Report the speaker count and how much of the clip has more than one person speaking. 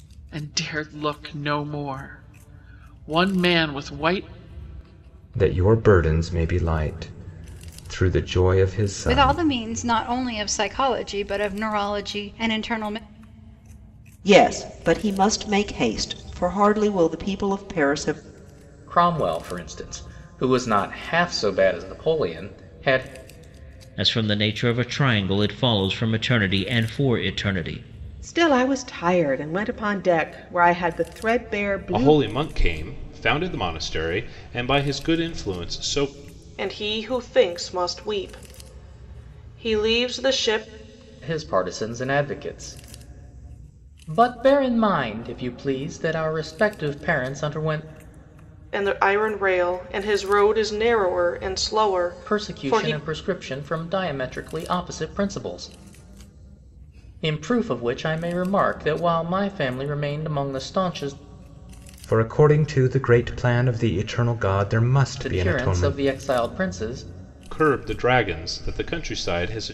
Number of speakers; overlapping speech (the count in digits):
9, about 3%